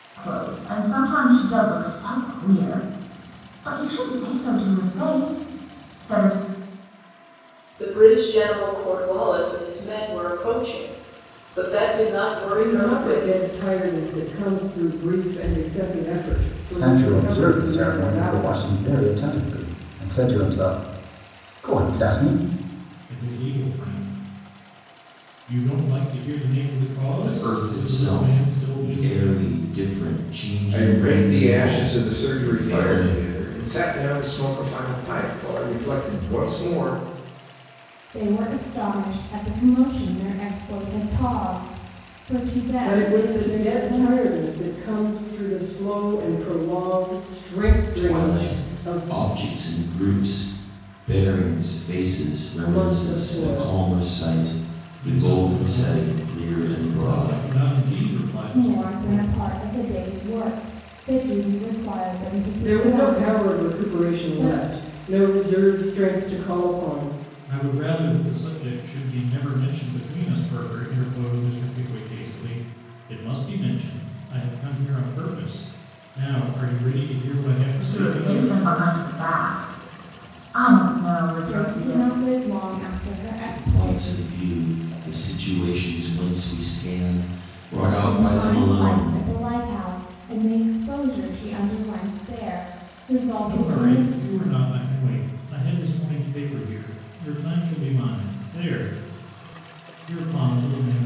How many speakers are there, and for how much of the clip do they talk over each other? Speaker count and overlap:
8, about 21%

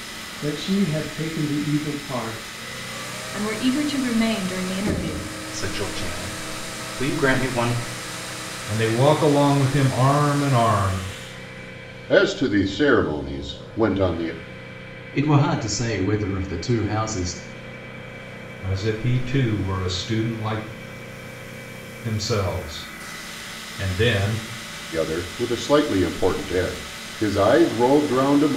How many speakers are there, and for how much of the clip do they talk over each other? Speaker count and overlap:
6, no overlap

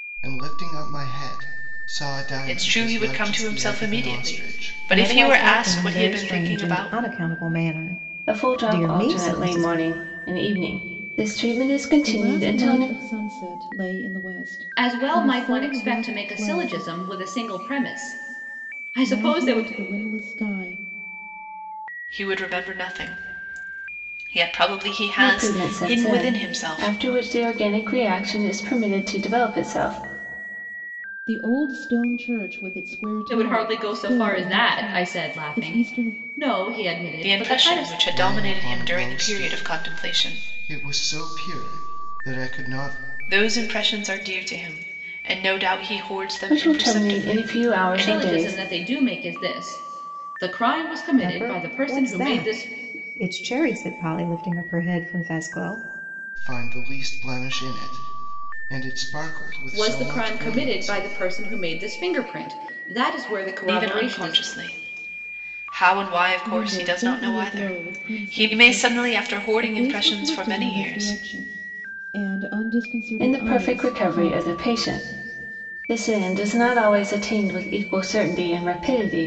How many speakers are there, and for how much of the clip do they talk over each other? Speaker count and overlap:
6, about 37%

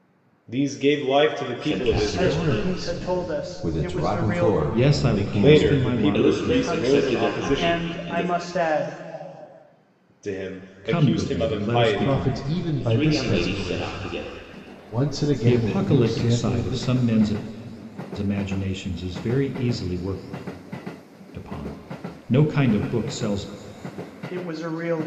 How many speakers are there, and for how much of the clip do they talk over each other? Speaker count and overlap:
6, about 44%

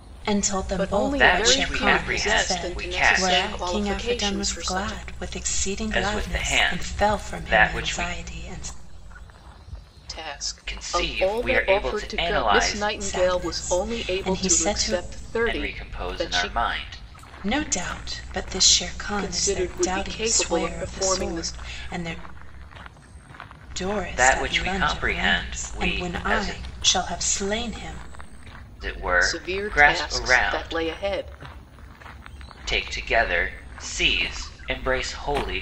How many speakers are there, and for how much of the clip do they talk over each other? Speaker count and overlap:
3, about 52%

